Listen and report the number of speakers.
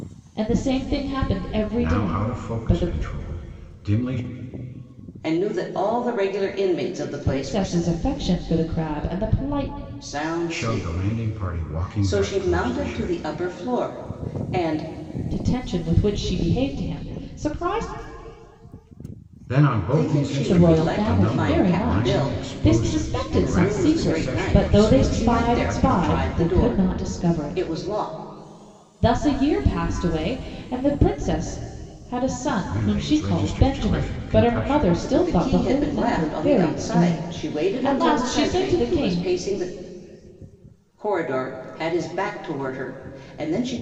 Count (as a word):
three